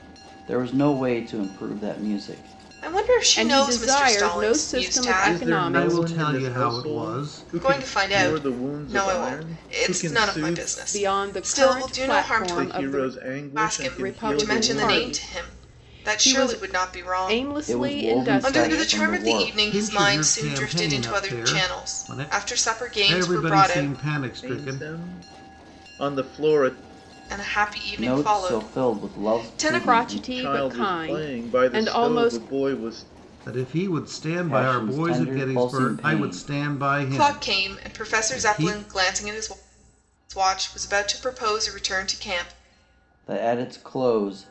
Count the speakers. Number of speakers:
five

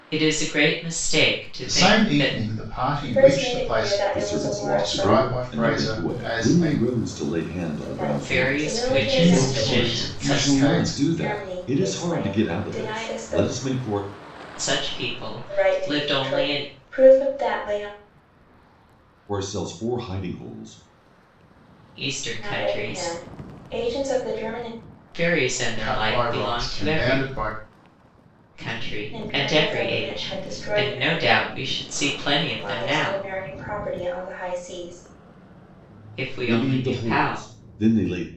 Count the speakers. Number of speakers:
four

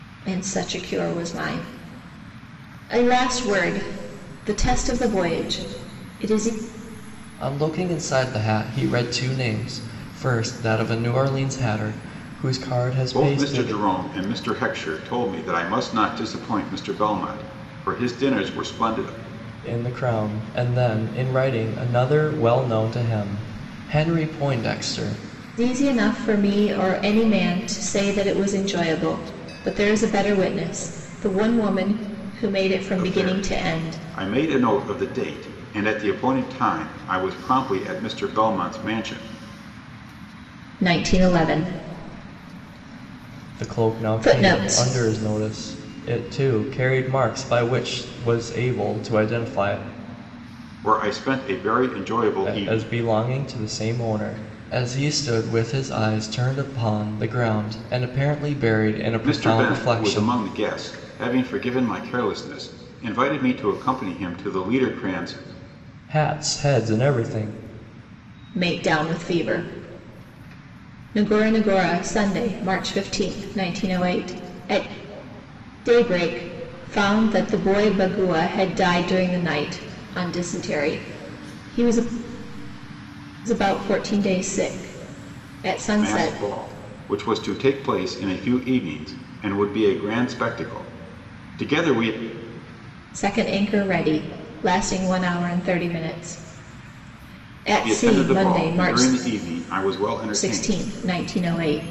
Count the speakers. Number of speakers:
three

